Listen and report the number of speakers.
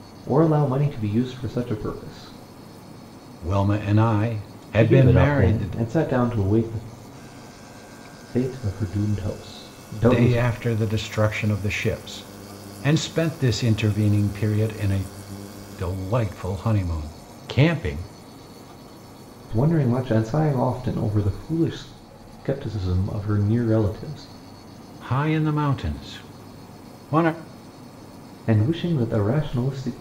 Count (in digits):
2